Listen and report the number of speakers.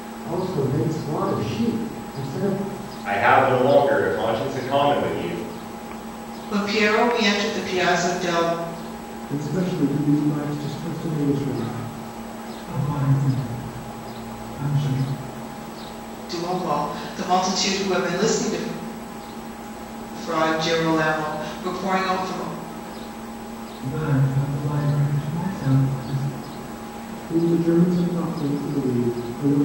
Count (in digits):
5